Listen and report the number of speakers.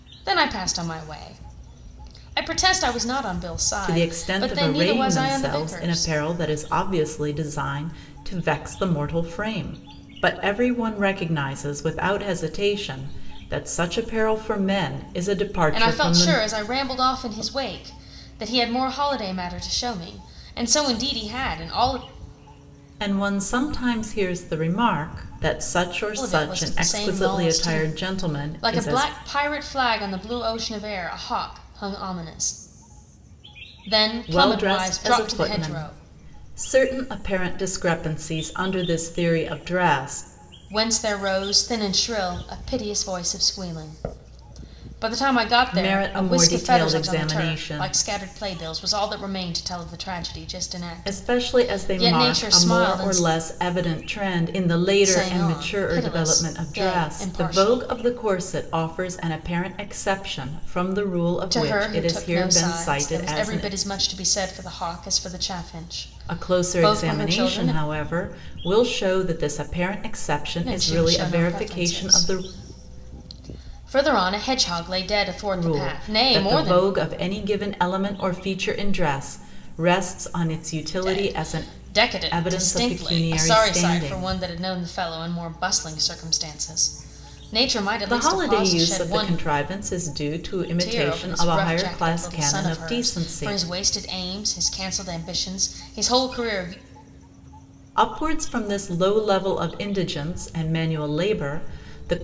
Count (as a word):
two